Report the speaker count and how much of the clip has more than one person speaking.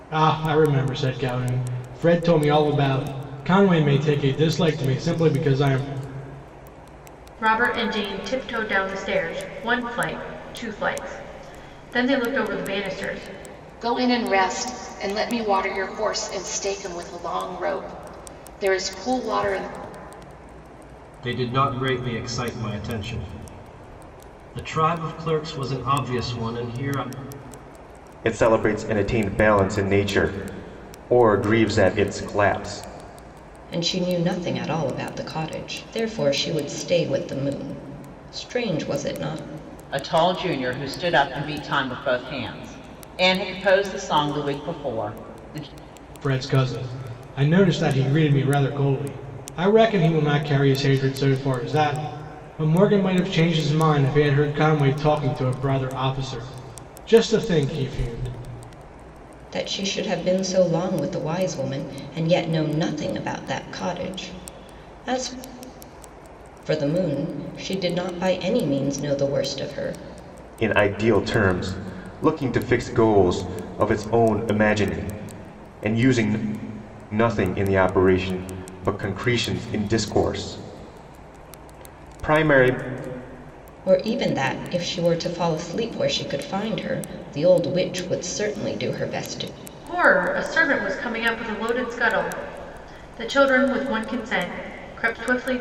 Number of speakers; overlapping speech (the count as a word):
seven, no overlap